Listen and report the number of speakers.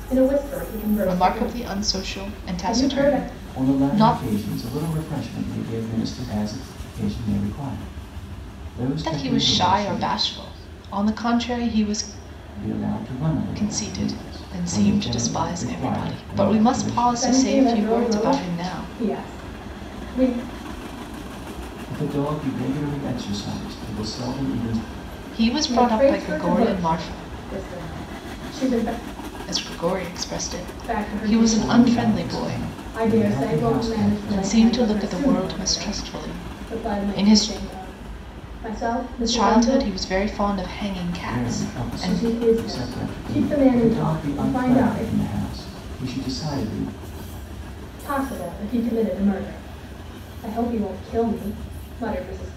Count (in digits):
3